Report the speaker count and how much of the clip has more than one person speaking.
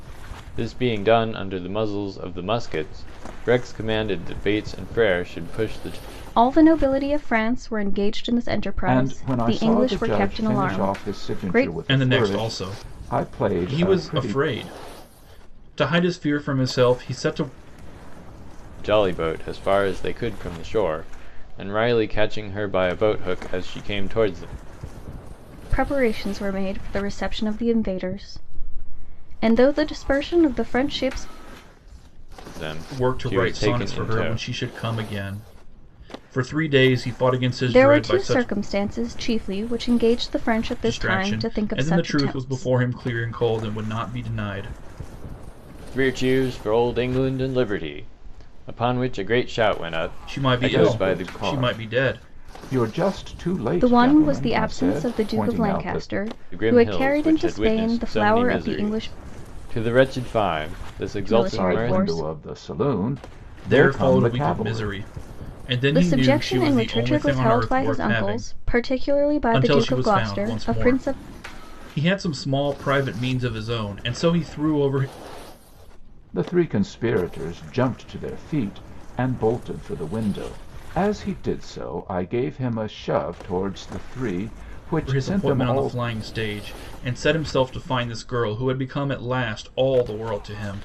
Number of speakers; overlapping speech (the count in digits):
4, about 27%